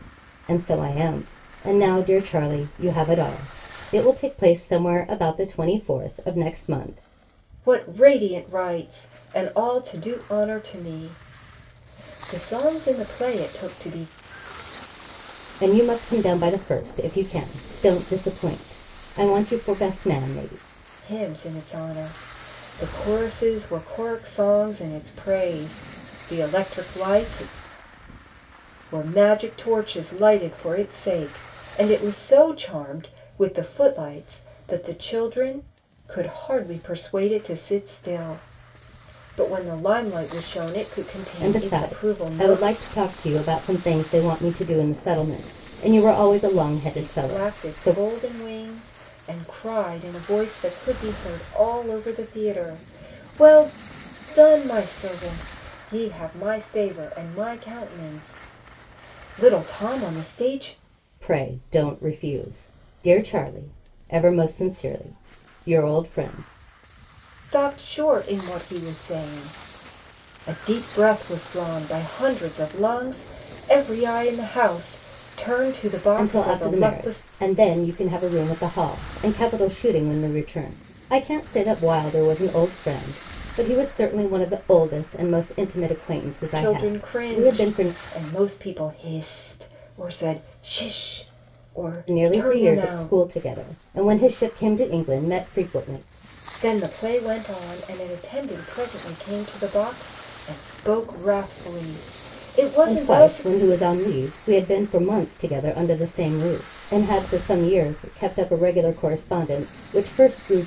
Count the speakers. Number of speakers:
two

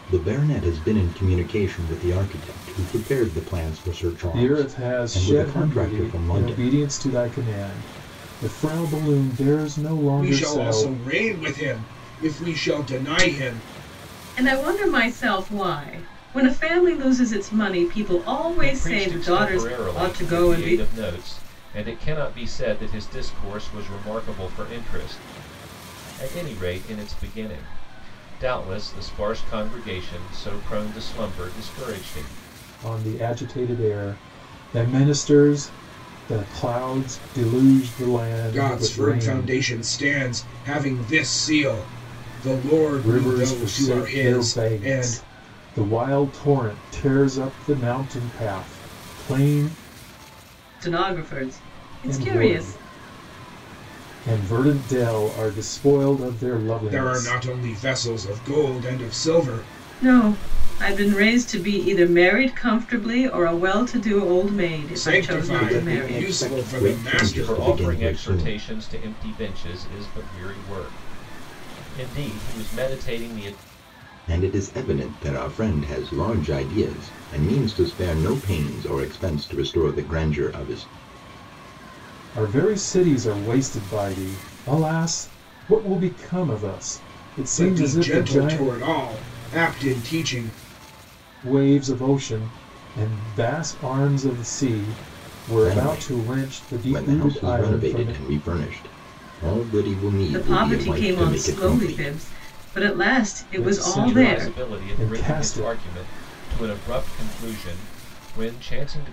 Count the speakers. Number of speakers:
five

